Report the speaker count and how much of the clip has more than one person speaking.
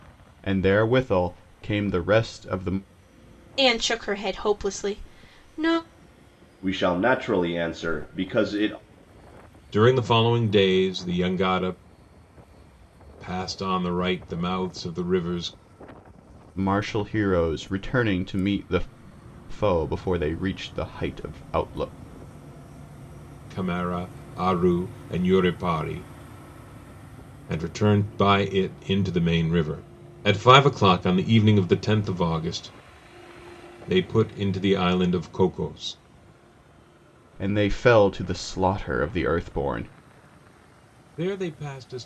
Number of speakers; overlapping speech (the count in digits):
4, no overlap